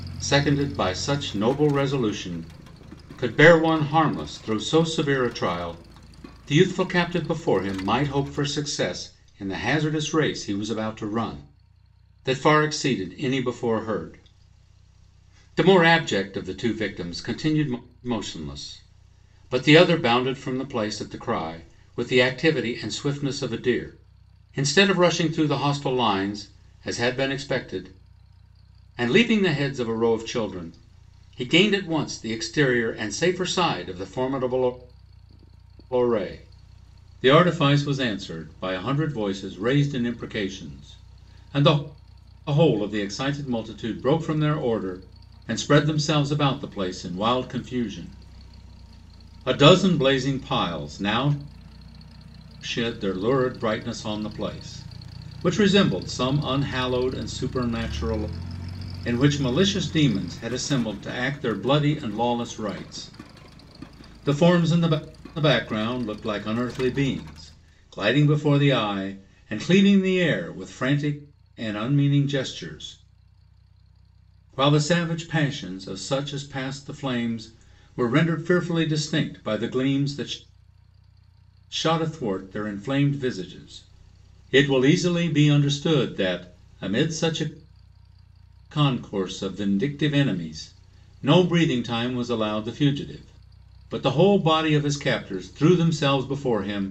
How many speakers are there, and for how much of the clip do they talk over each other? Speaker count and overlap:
1, no overlap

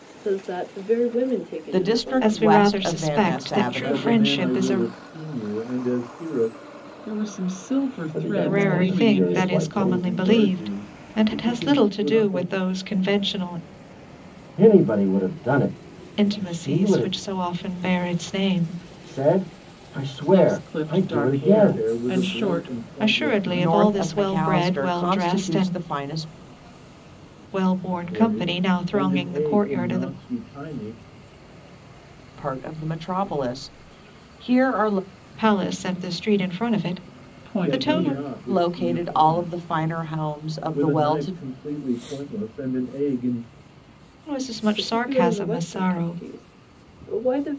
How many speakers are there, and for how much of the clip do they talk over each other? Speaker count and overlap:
6, about 43%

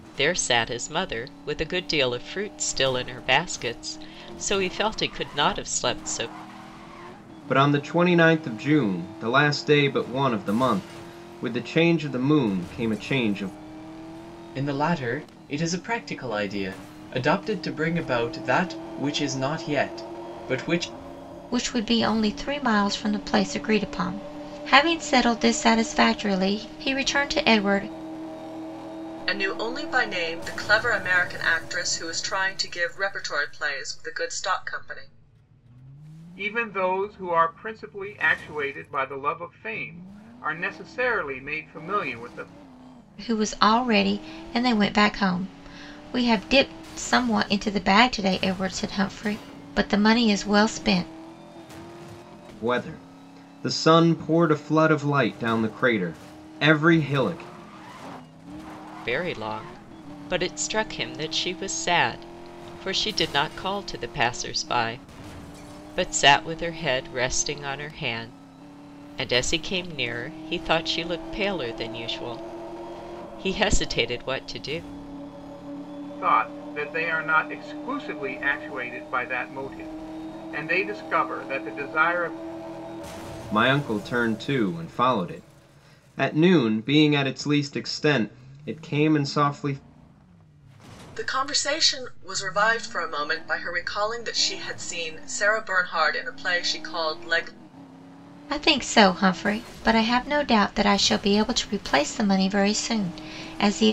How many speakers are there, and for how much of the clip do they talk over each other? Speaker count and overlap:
6, no overlap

